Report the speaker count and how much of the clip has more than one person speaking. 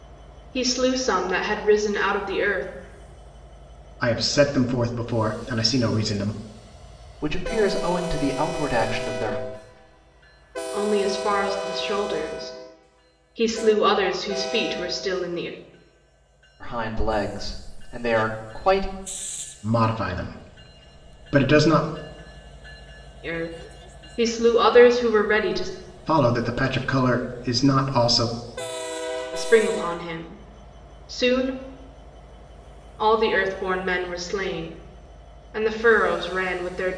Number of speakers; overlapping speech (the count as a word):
three, no overlap